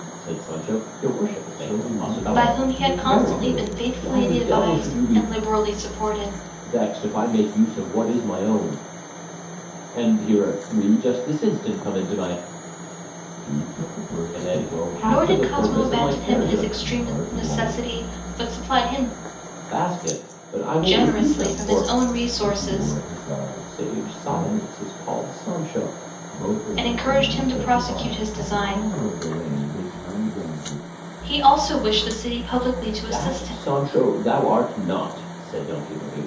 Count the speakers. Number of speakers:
3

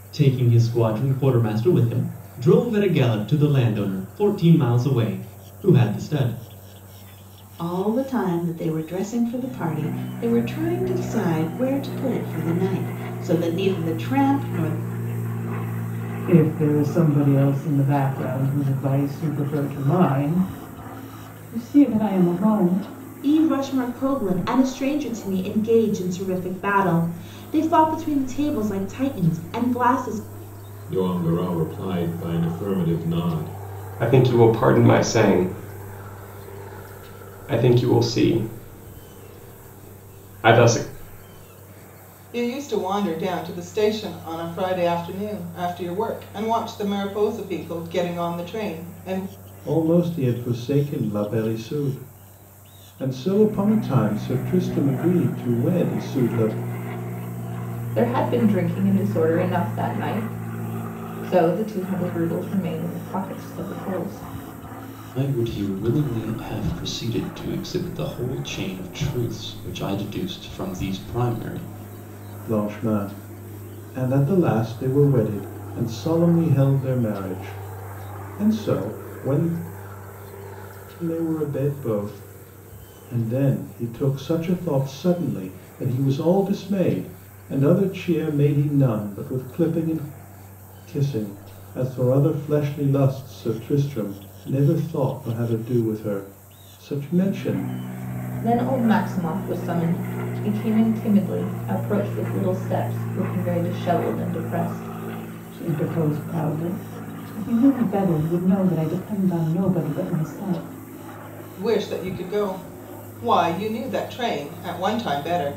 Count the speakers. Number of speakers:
10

